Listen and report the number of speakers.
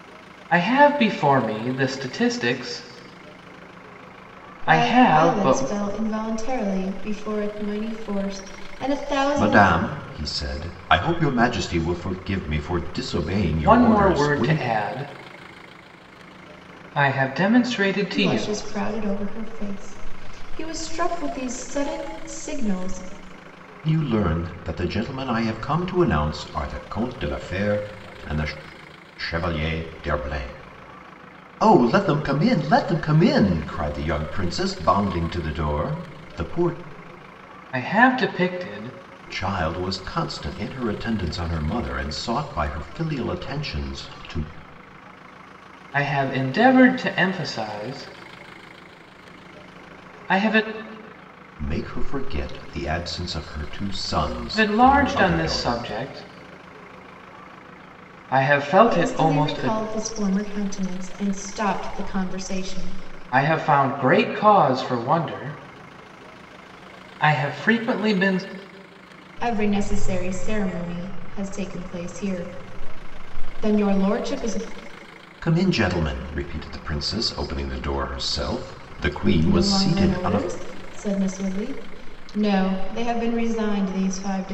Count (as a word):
three